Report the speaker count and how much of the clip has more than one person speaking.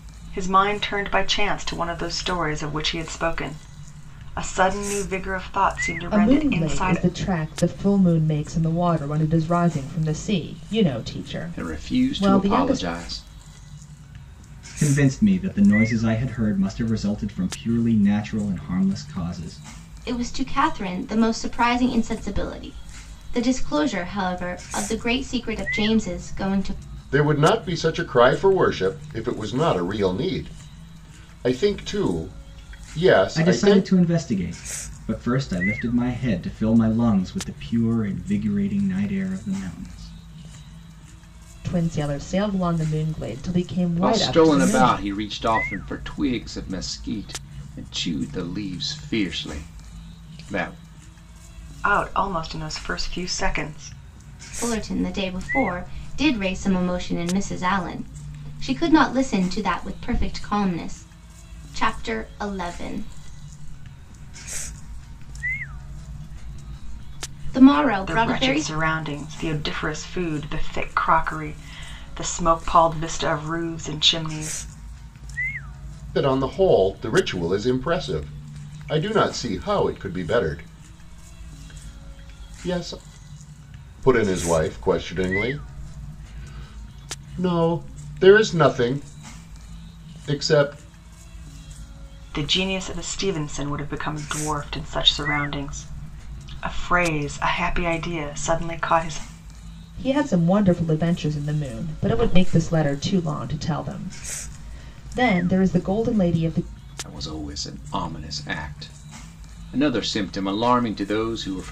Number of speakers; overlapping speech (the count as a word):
six, about 4%